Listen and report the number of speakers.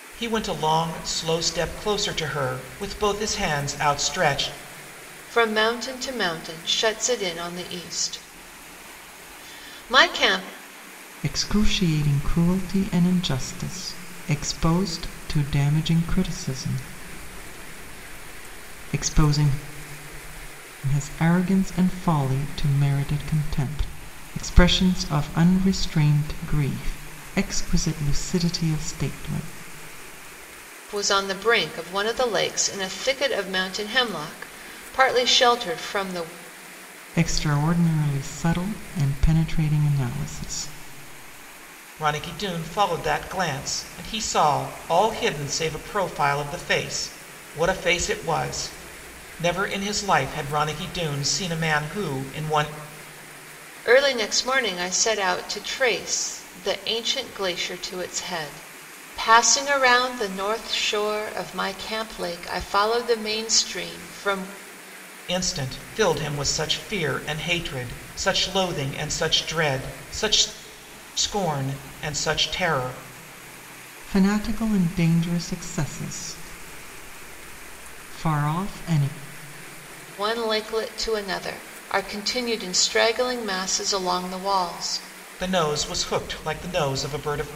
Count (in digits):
3